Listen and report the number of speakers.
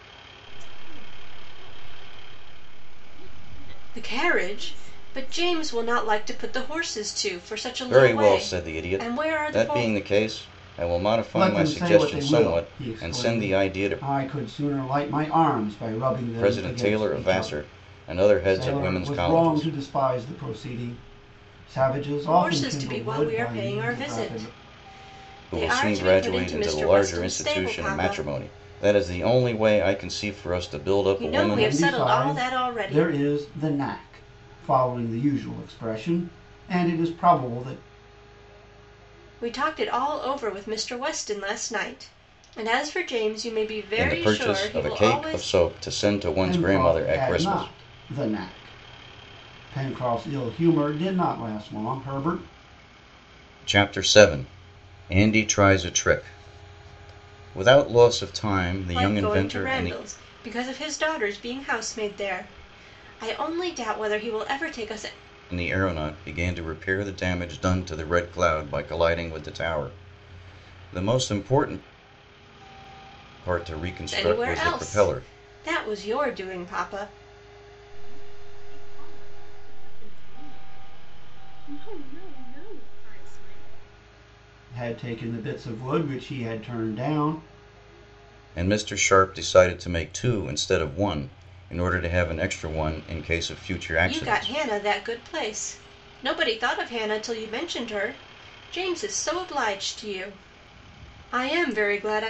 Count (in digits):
4